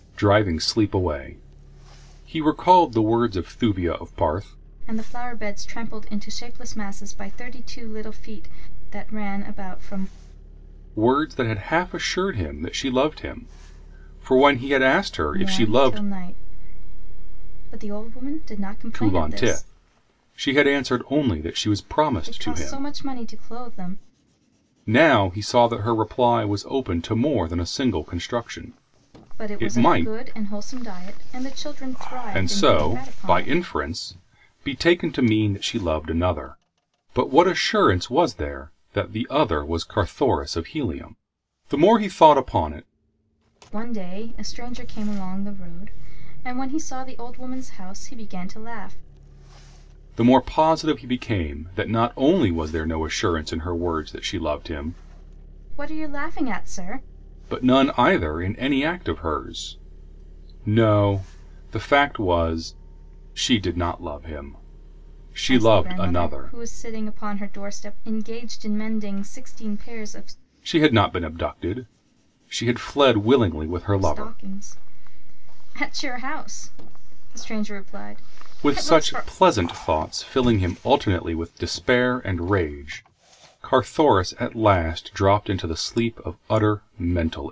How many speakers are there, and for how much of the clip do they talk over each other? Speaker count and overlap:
two, about 8%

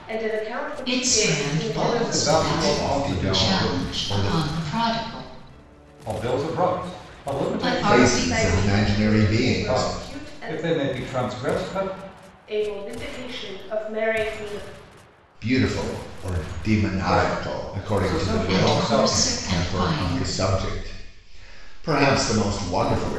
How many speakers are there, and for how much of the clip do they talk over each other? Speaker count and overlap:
four, about 43%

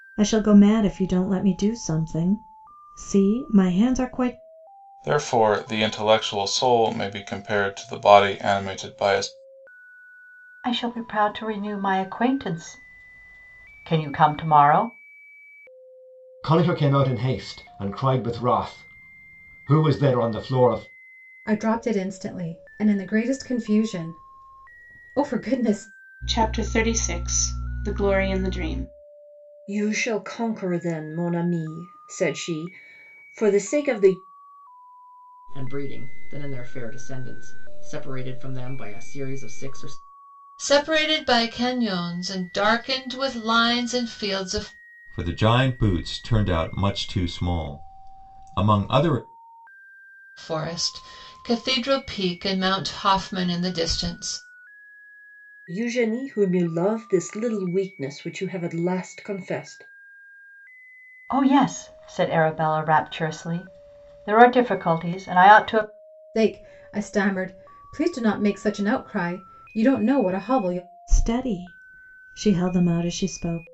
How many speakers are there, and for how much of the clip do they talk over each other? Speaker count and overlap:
ten, no overlap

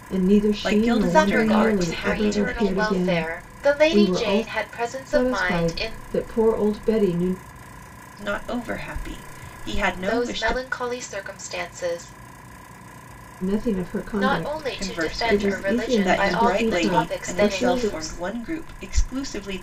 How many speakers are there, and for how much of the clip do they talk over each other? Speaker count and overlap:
three, about 49%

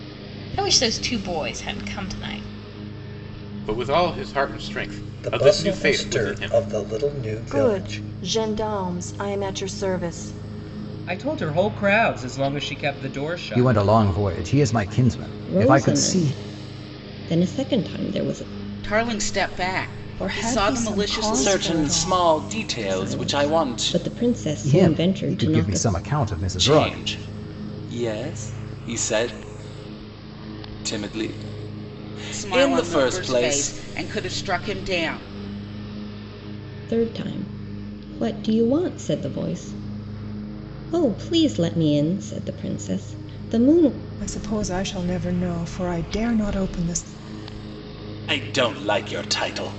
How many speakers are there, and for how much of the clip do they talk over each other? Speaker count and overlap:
ten, about 19%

